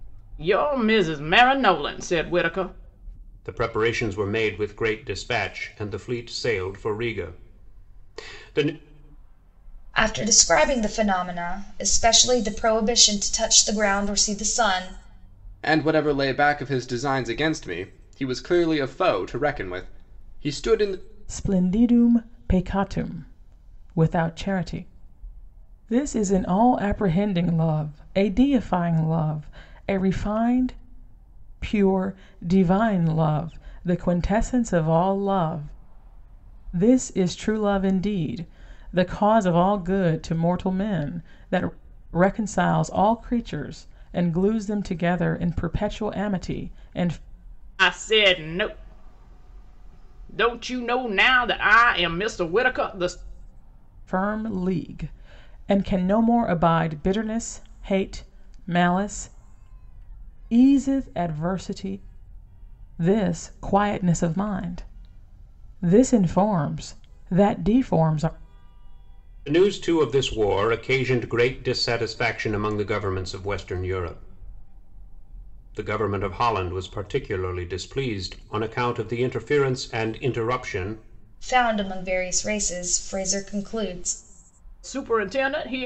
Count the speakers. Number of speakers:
five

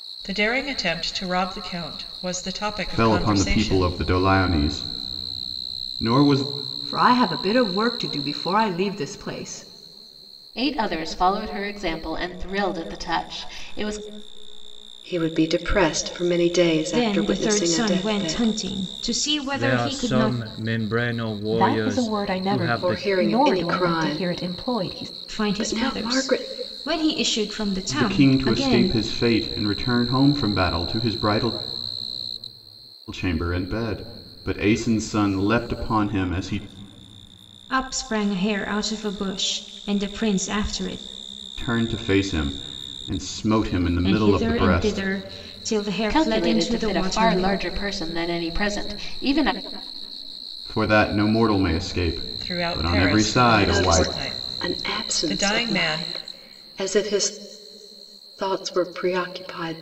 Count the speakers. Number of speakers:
eight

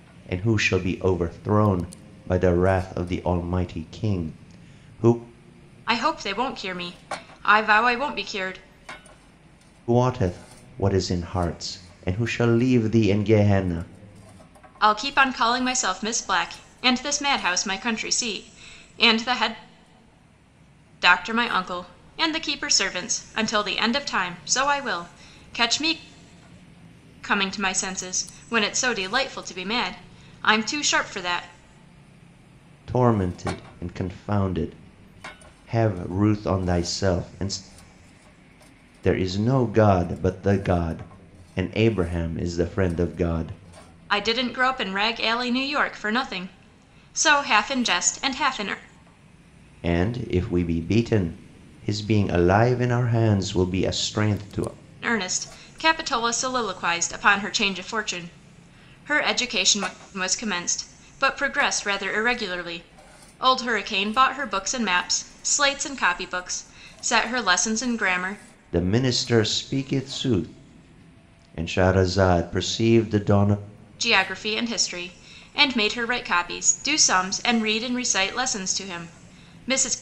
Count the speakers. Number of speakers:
two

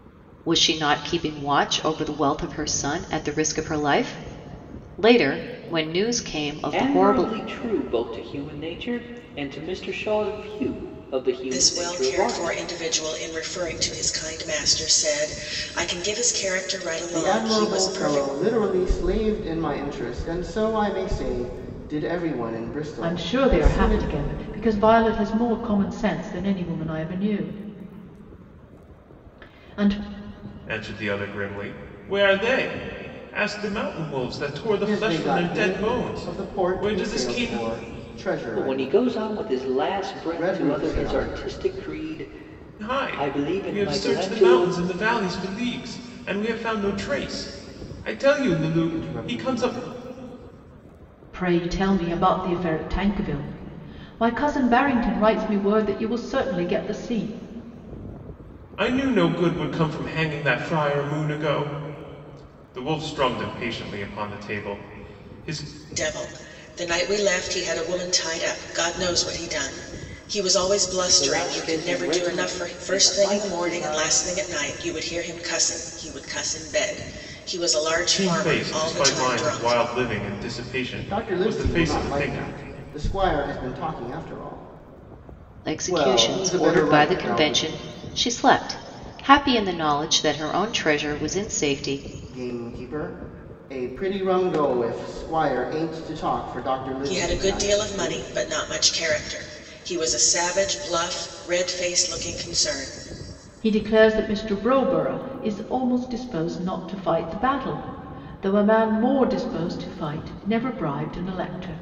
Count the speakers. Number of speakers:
six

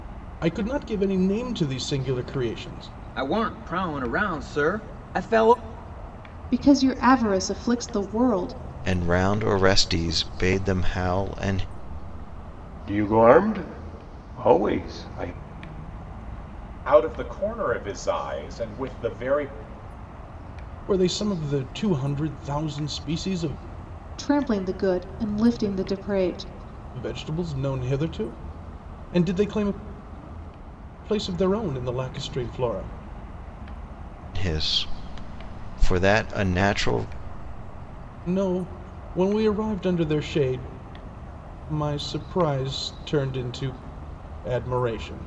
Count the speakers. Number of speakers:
six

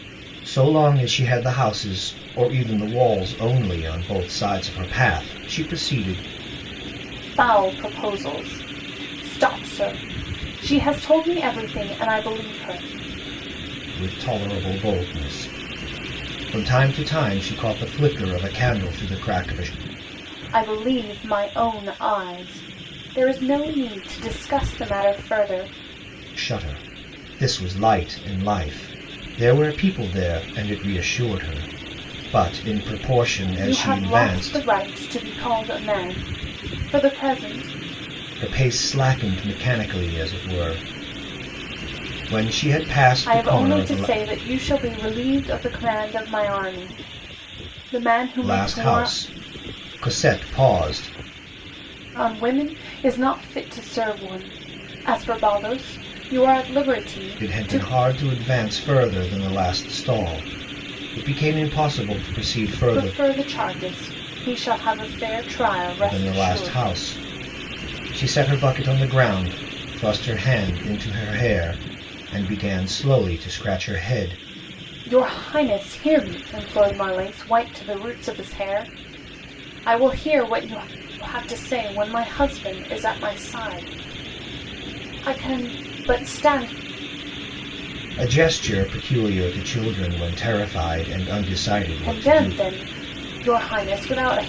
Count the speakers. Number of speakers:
two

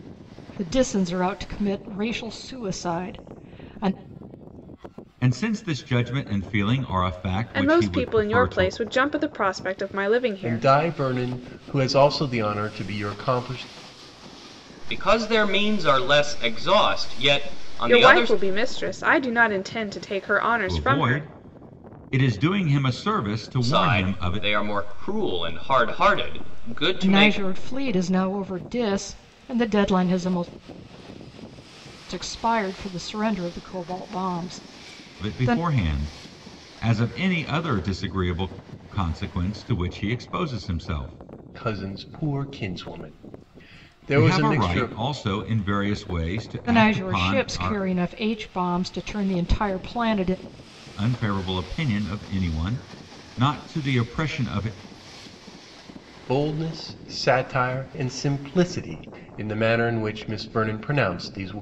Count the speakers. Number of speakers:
five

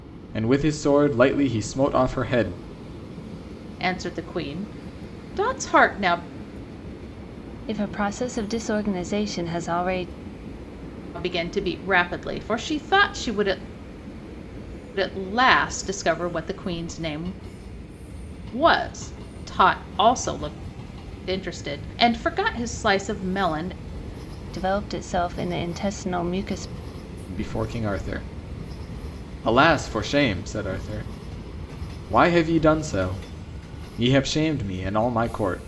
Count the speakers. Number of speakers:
three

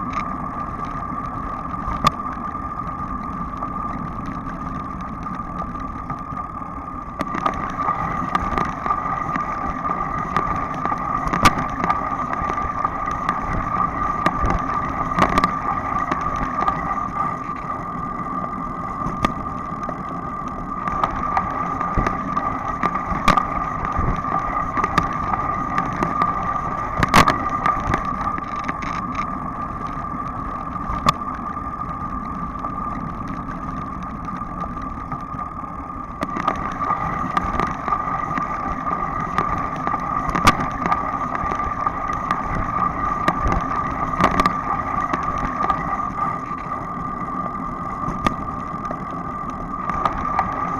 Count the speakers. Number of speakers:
zero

